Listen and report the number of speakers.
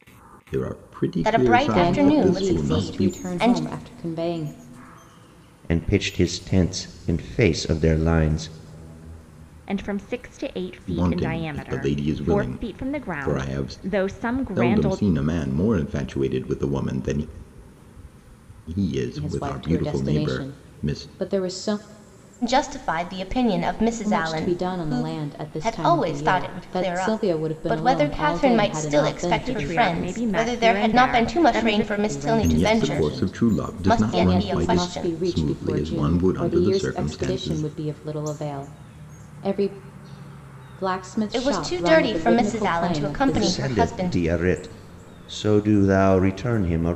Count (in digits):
5